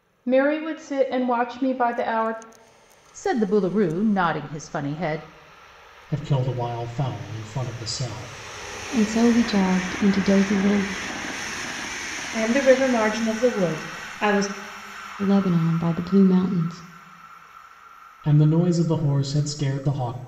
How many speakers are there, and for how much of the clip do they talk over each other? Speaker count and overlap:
5, no overlap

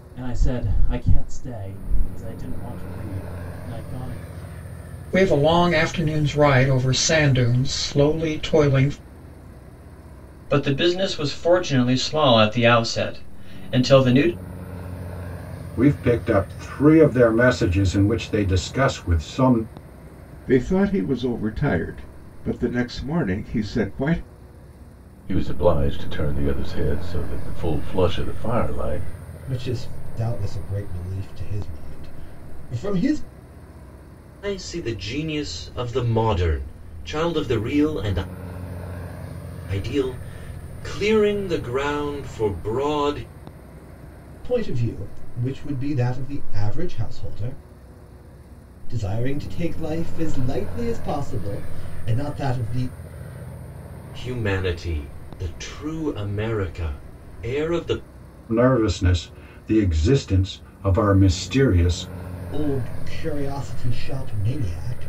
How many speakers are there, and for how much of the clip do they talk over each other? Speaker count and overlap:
8, no overlap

